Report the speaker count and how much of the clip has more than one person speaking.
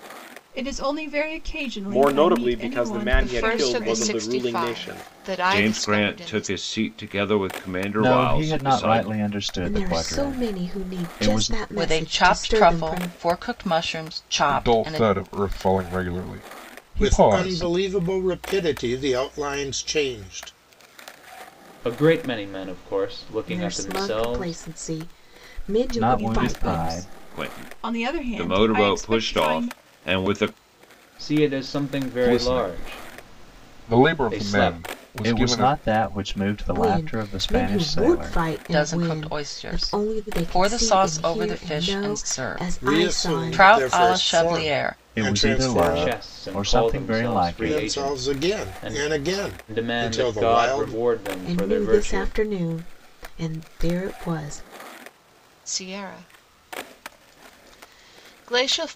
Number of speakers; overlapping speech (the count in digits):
10, about 55%